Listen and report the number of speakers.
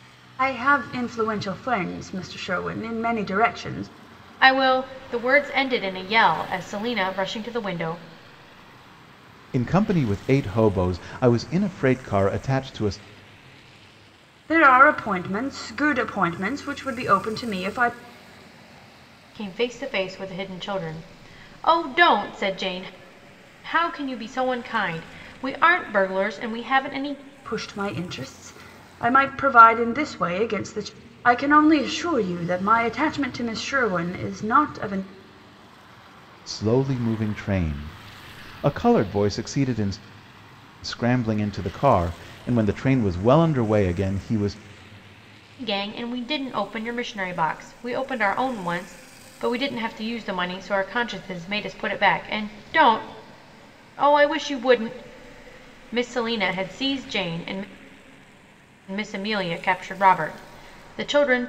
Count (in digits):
3